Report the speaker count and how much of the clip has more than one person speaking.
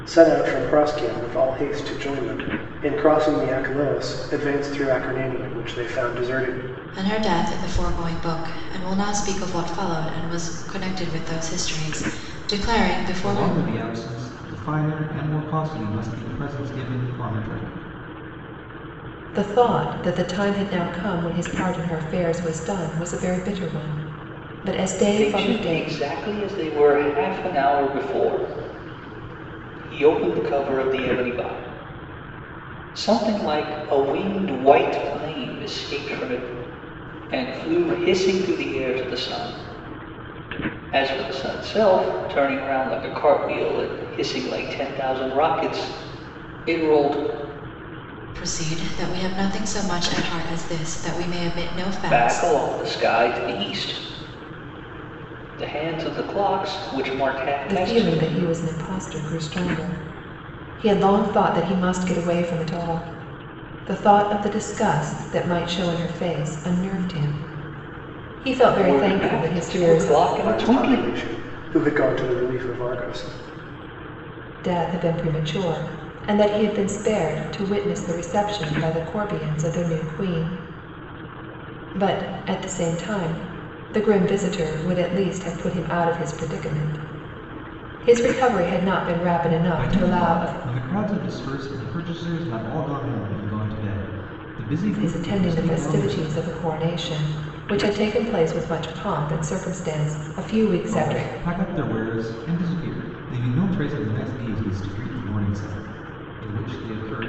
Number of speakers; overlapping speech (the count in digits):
5, about 7%